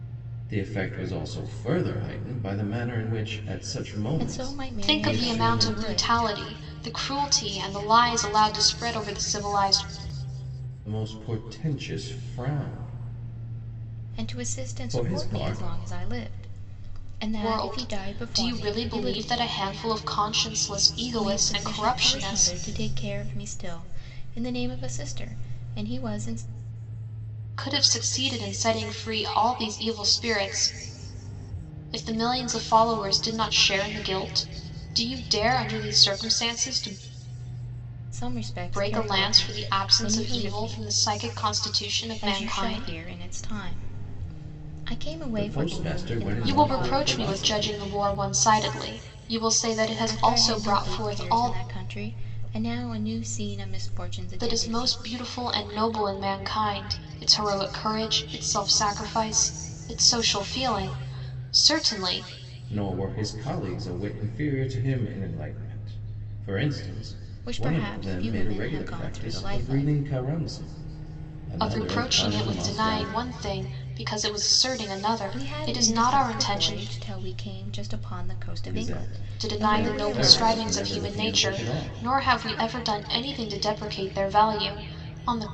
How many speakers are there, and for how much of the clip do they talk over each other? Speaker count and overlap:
three, about 28%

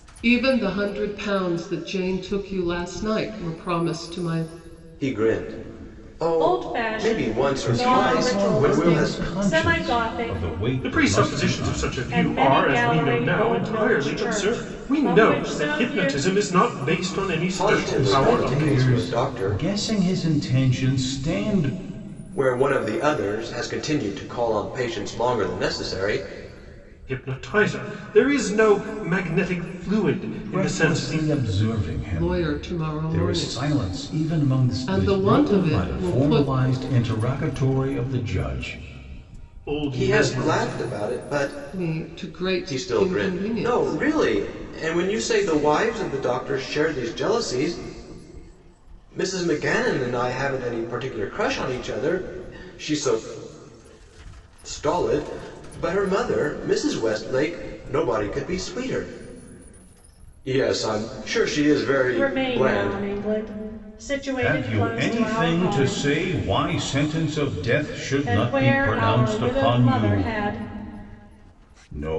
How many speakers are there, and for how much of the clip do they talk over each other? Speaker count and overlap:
five, about 35%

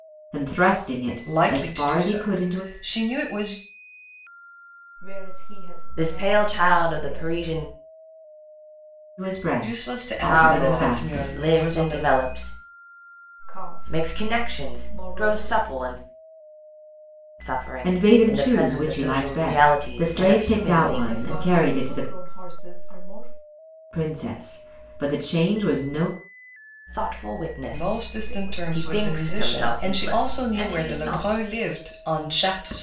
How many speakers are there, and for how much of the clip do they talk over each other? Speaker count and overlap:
four, about 46%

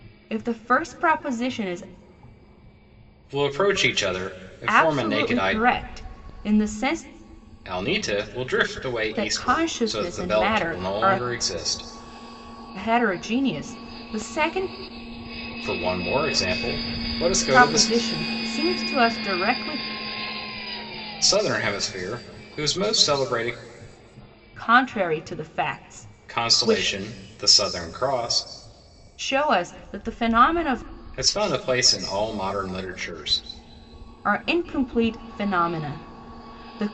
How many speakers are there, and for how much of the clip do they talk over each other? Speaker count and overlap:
two, about 12%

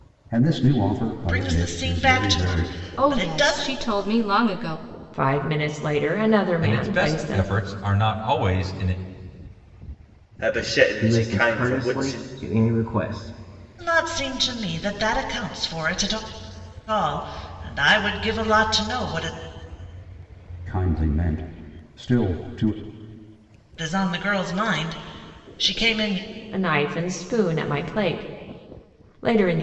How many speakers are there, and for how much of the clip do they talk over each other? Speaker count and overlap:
seven, about 15%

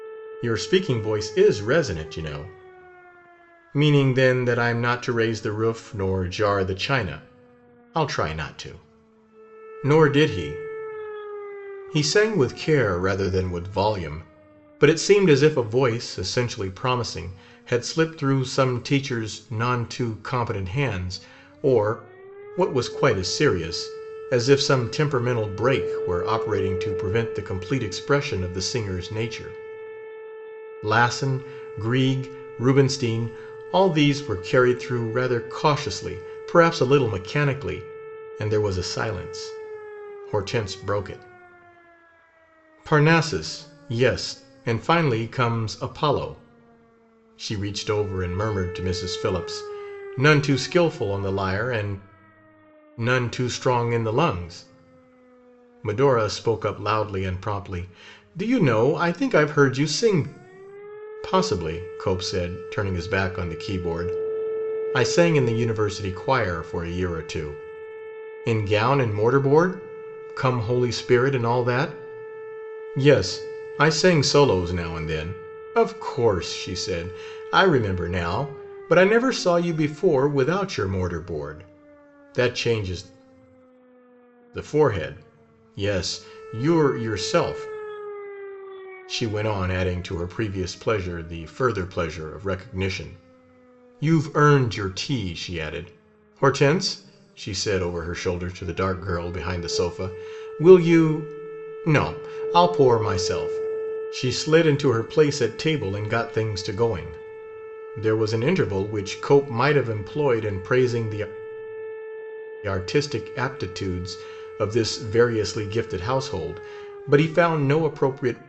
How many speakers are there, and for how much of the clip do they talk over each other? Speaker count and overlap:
one, no overlap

